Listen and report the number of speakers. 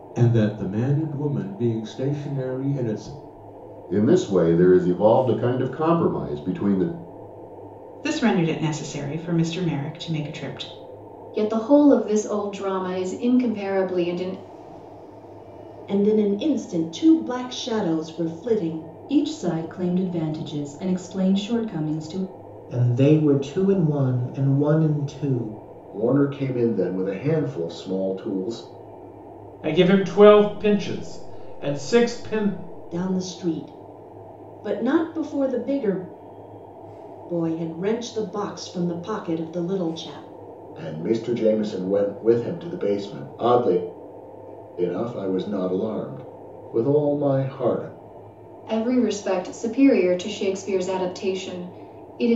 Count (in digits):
9